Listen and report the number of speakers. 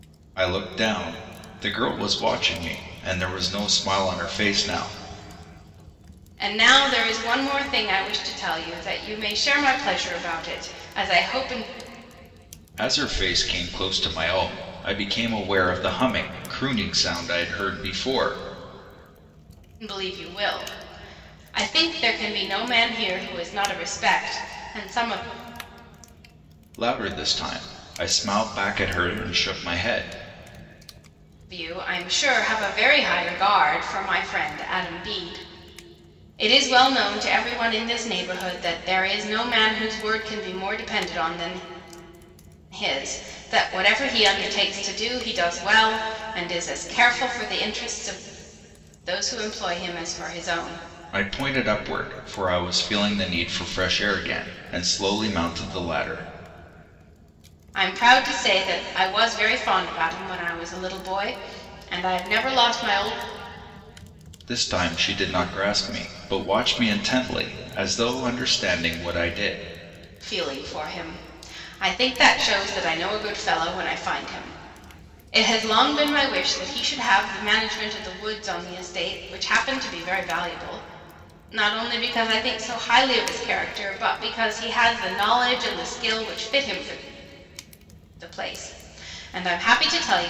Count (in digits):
2